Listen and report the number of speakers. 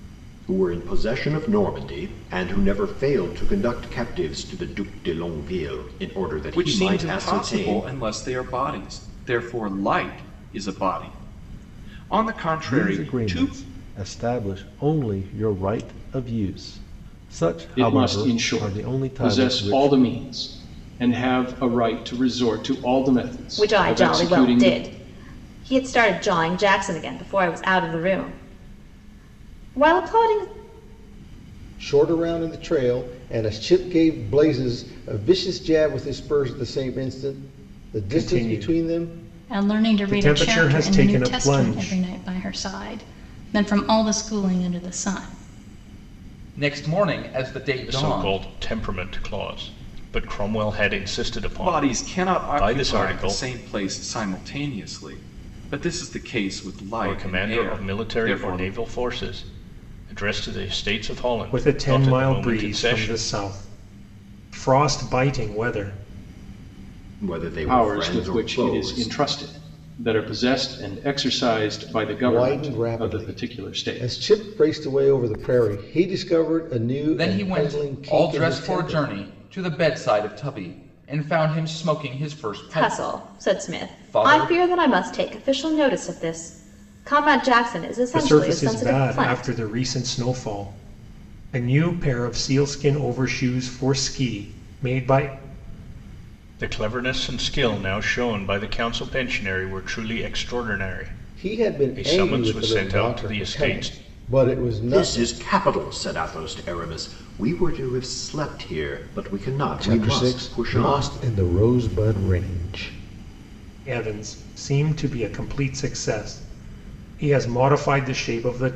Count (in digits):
10